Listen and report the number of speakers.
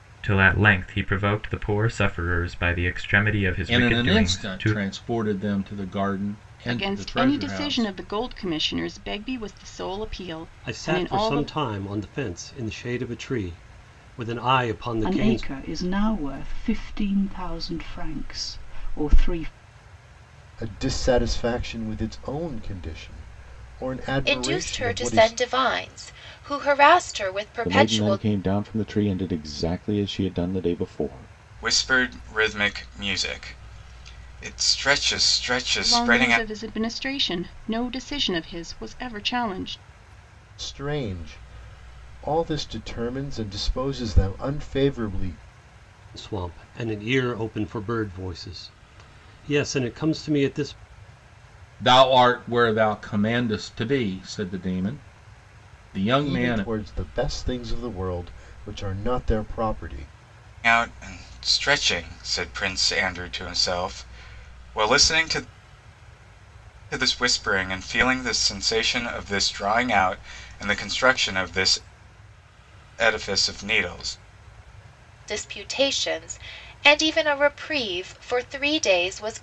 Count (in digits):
9